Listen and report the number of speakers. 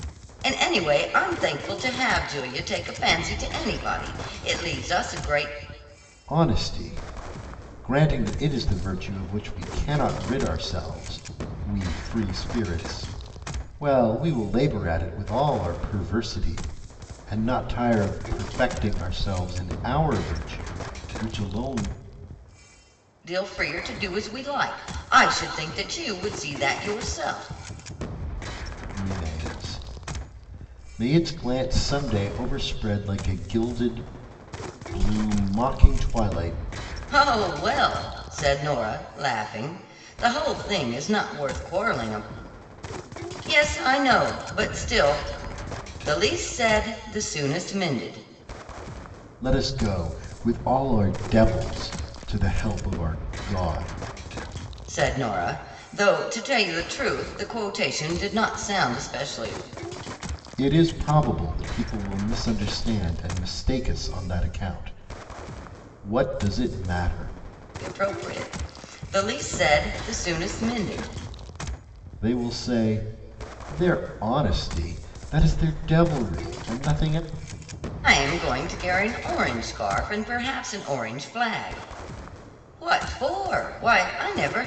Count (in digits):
2